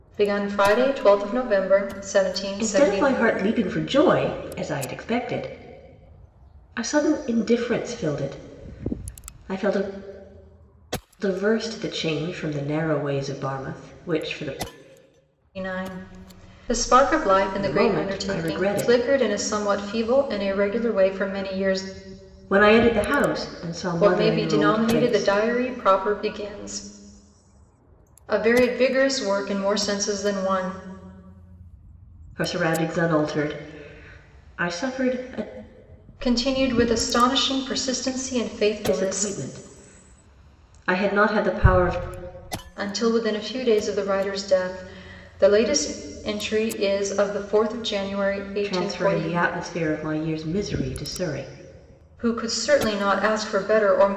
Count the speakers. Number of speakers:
2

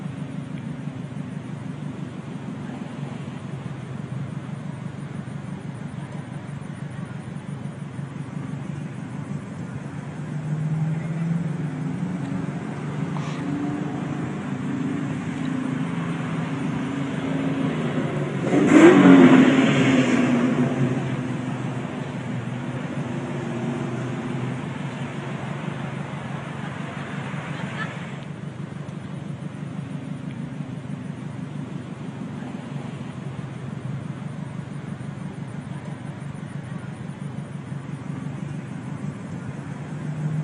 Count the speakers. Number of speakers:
0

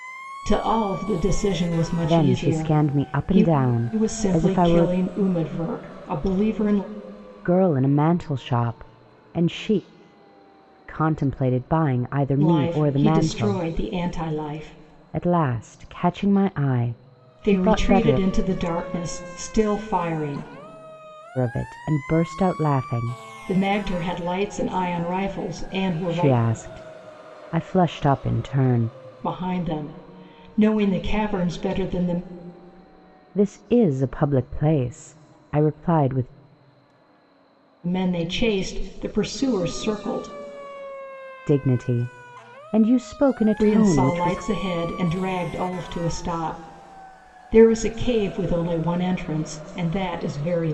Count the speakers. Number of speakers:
2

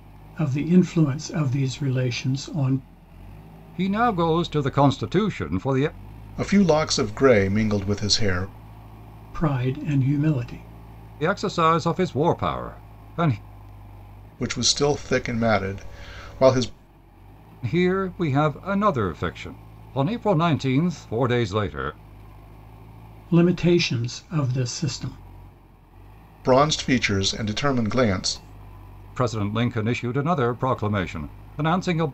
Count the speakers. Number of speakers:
3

